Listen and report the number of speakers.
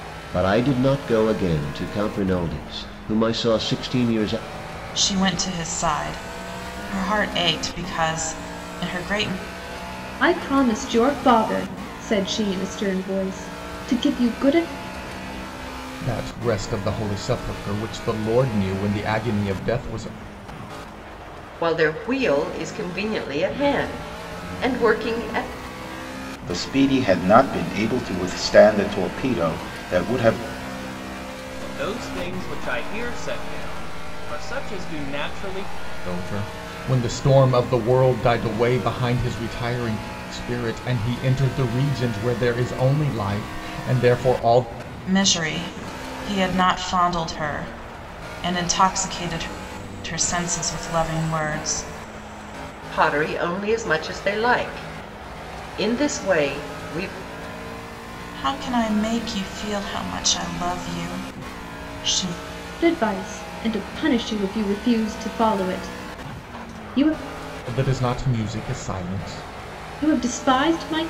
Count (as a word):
seven